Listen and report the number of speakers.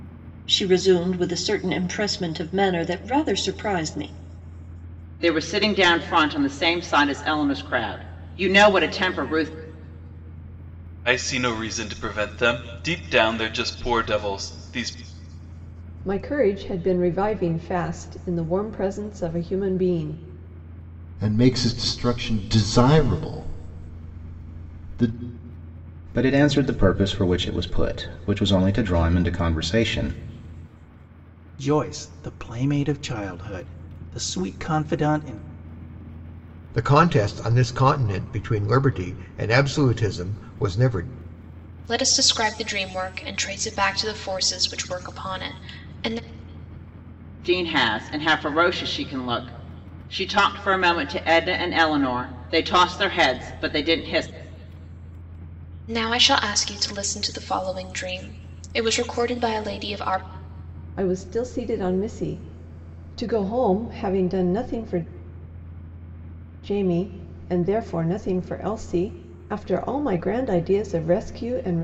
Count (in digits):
9